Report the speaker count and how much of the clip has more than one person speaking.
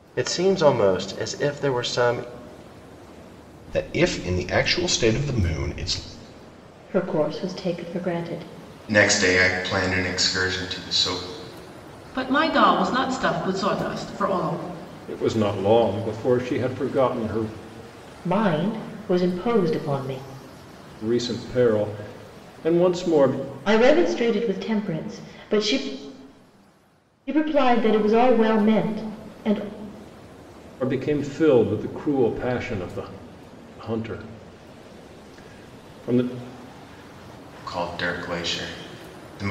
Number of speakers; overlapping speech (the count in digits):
6, no overlap